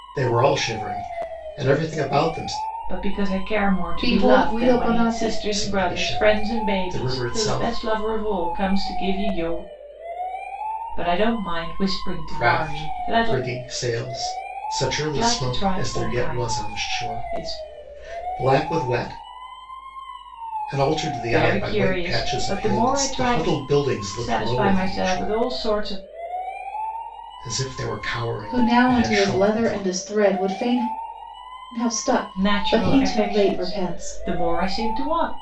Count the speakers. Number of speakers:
3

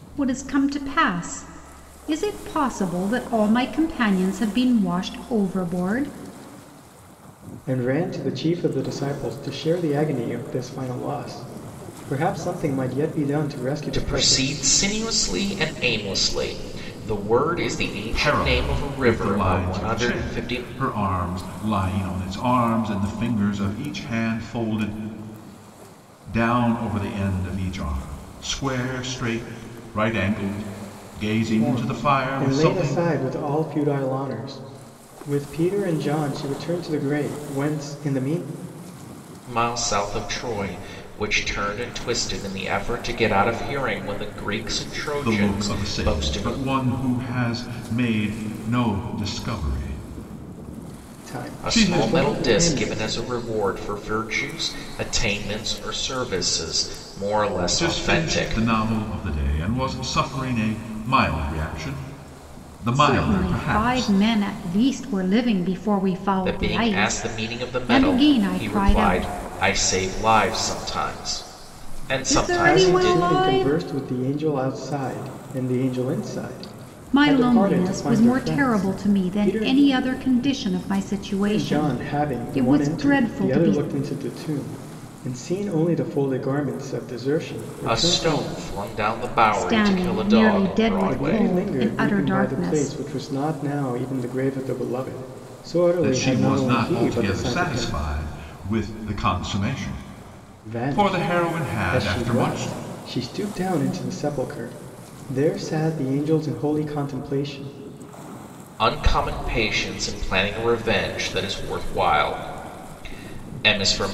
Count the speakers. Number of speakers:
4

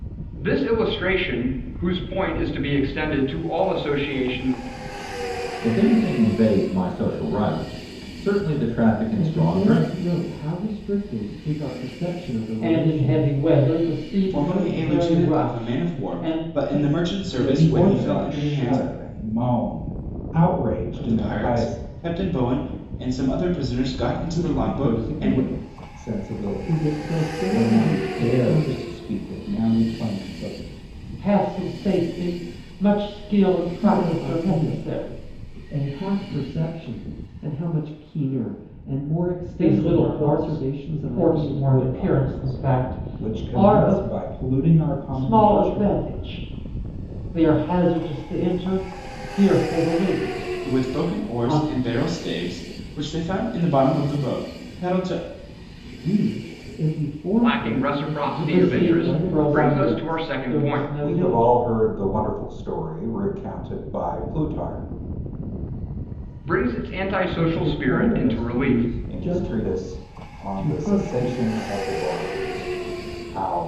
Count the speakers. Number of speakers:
6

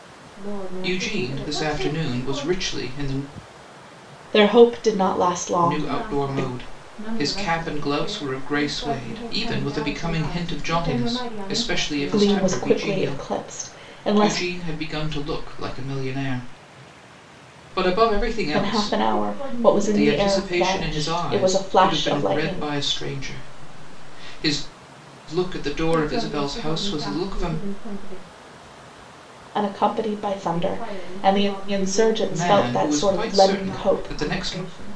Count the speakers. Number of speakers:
3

